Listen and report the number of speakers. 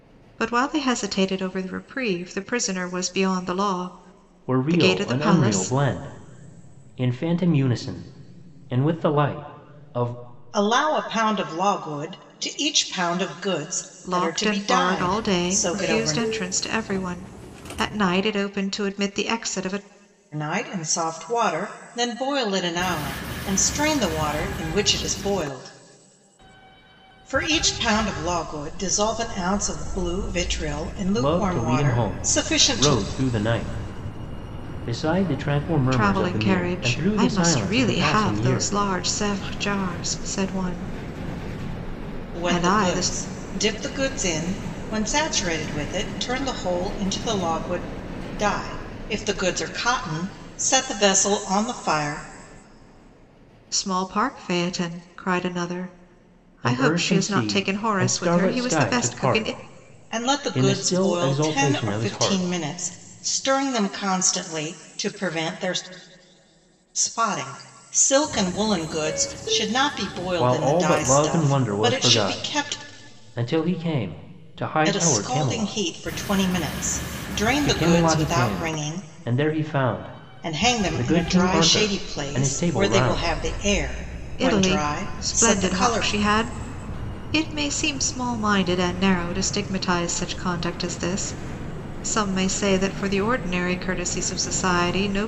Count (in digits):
3